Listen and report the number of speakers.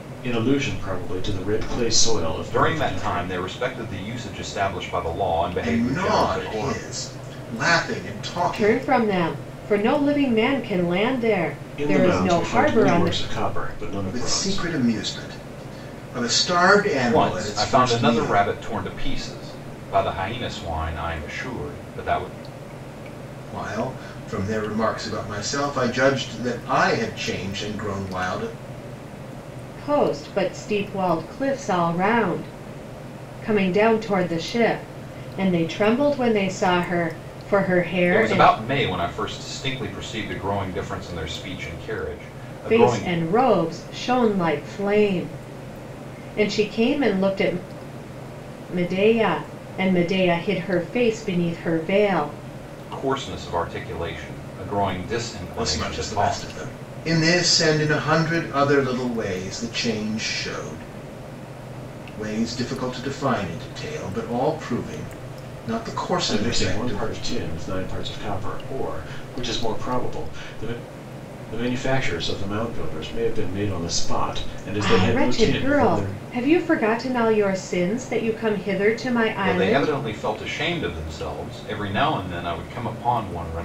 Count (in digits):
4